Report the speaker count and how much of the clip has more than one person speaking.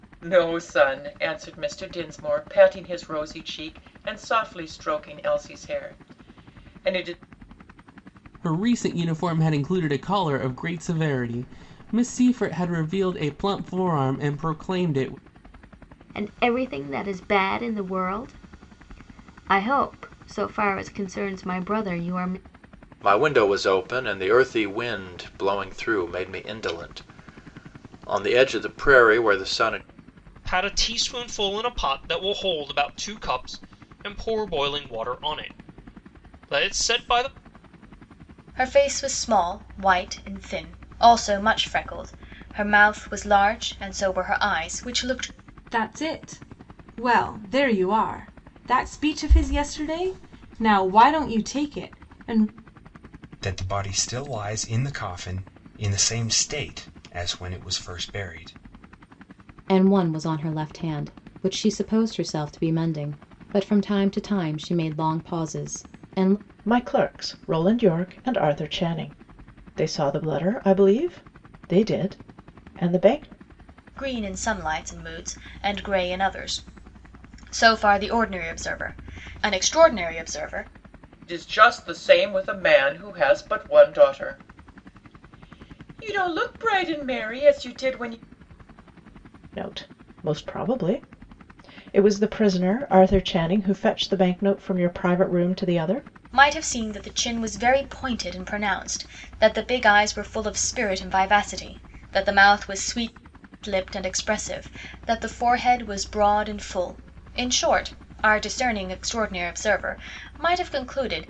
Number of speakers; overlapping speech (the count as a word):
ten, no overlap